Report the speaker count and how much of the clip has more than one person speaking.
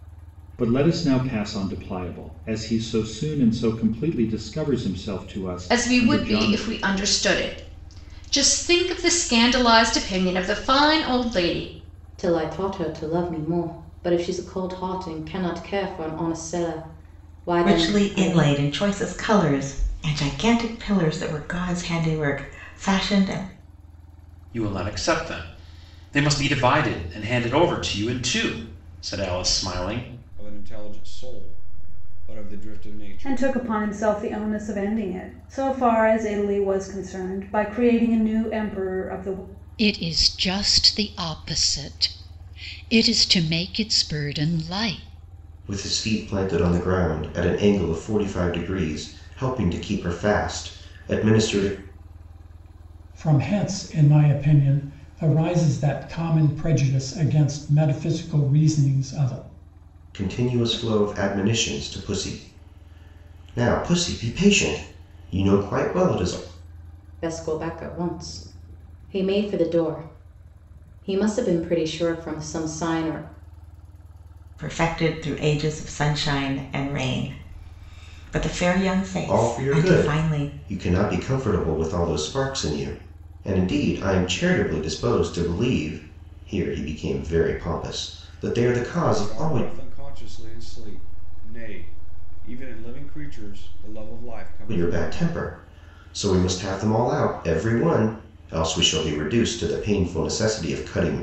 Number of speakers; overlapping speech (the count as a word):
ten, about 4%